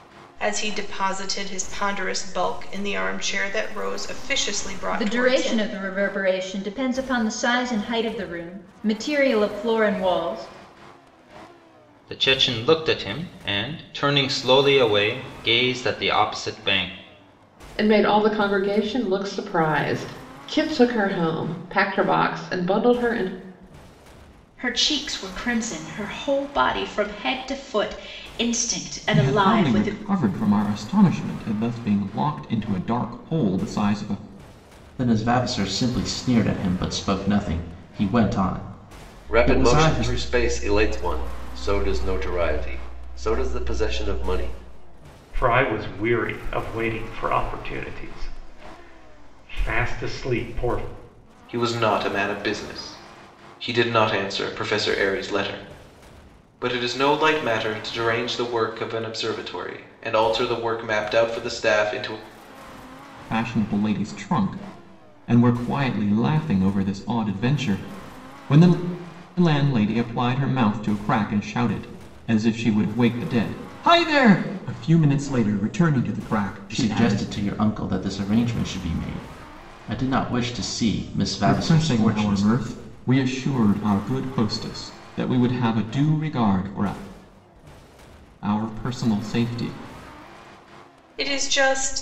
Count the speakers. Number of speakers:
ten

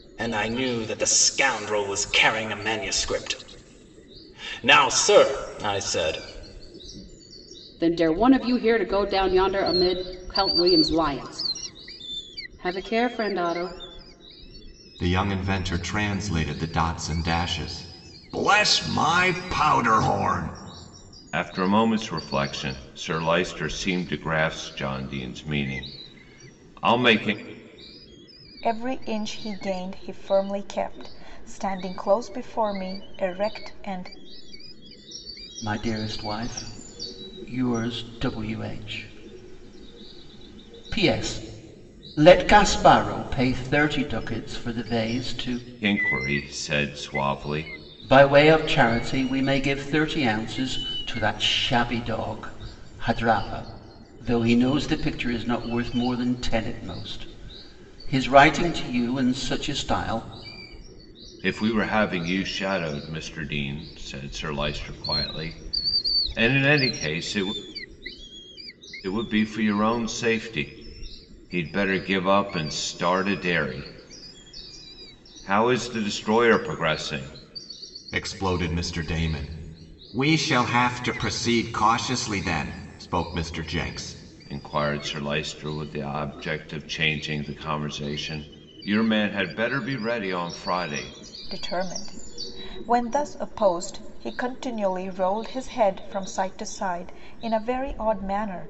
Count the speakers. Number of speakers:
six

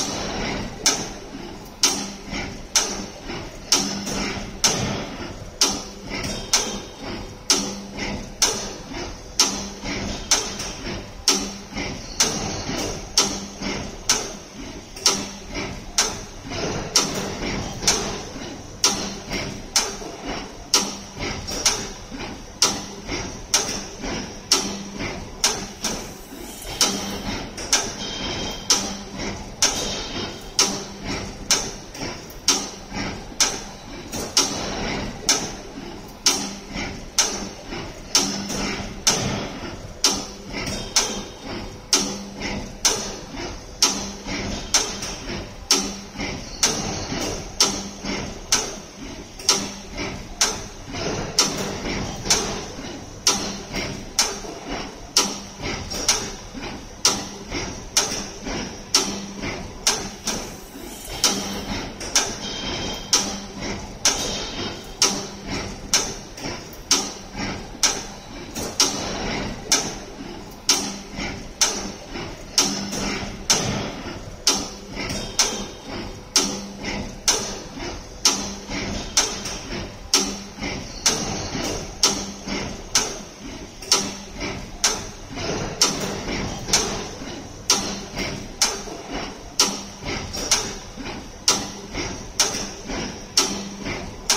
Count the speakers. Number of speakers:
zero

